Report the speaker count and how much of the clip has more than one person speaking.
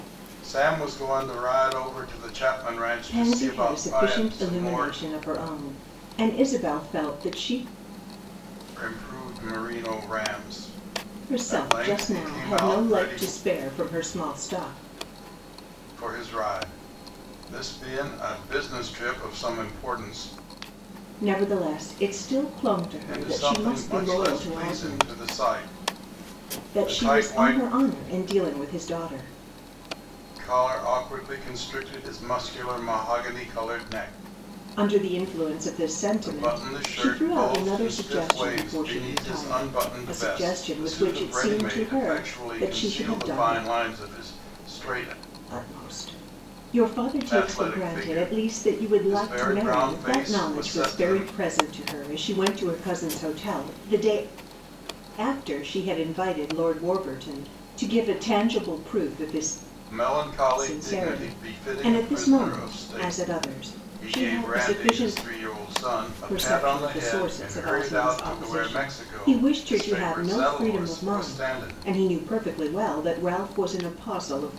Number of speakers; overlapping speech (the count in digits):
2, about 37%